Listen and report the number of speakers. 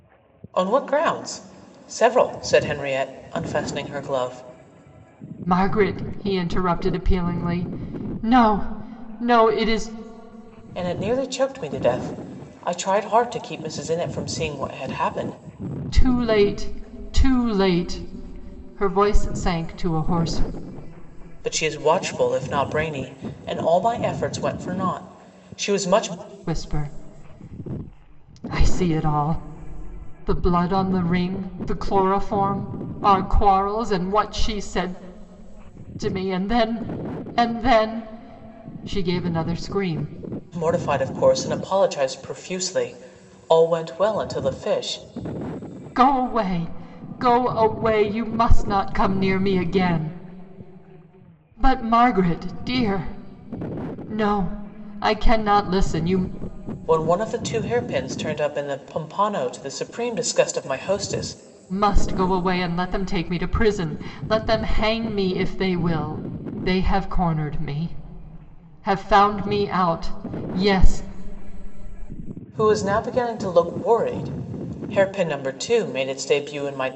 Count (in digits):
2